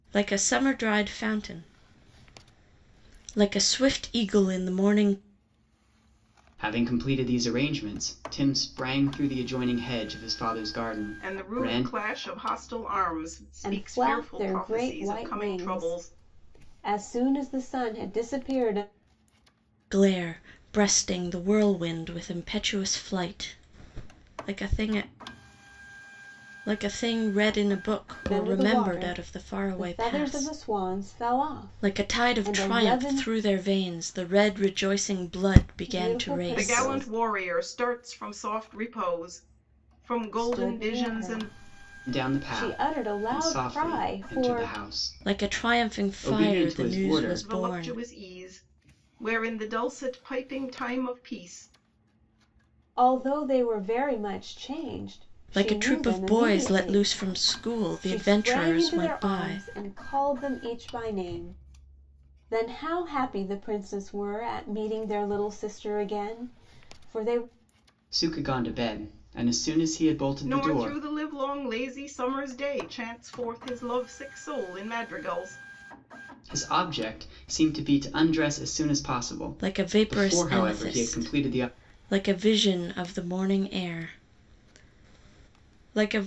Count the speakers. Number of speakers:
4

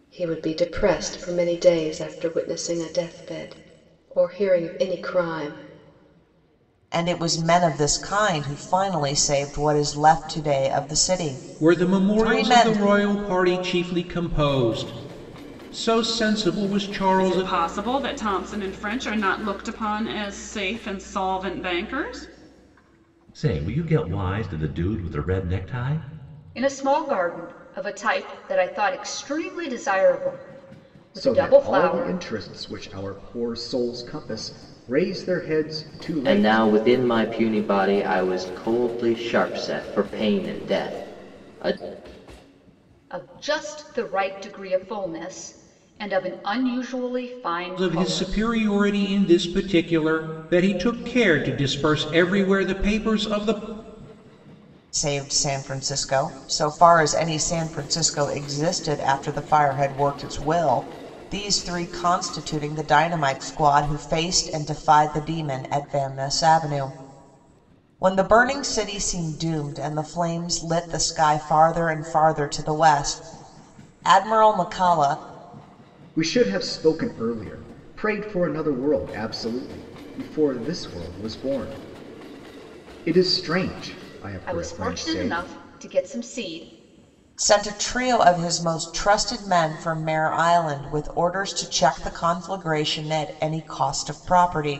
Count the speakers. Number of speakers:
8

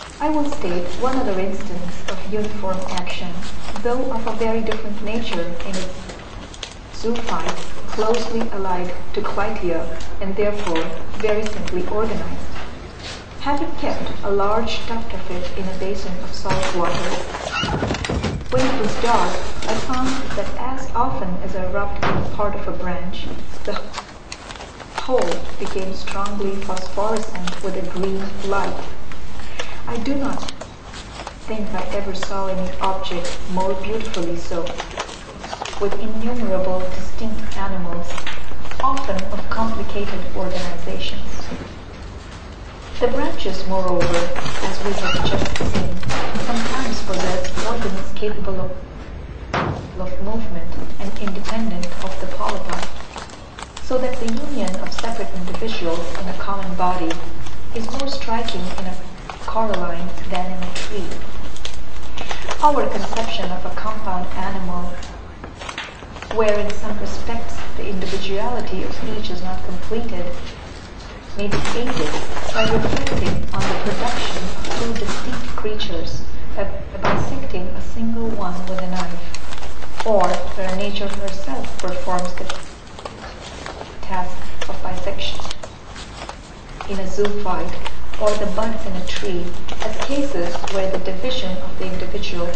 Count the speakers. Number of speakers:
1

